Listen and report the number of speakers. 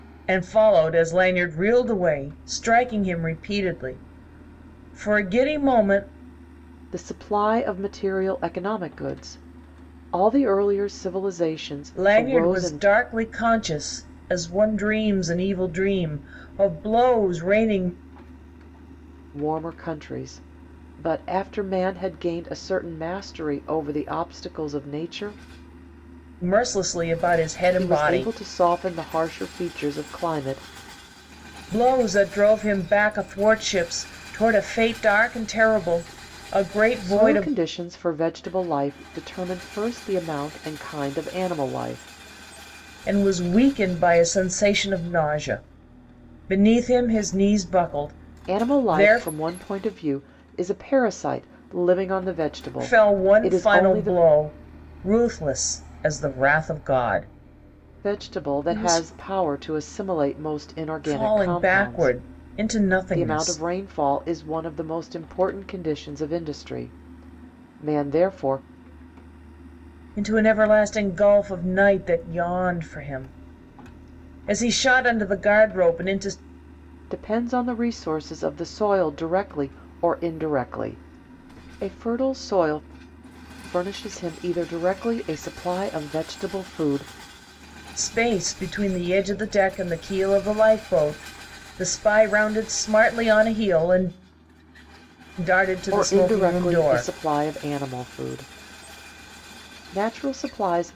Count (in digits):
2